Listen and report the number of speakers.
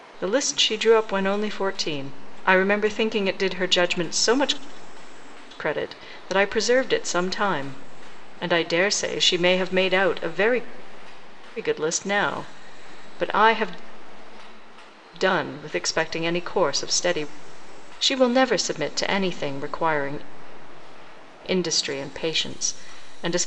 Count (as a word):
one